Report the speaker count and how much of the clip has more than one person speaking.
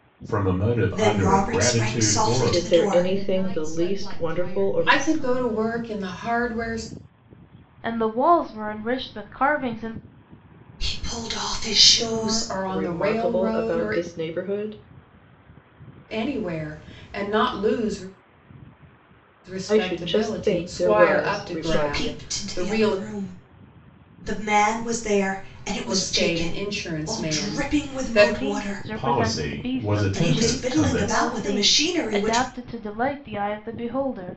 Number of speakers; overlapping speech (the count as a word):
six, about 46%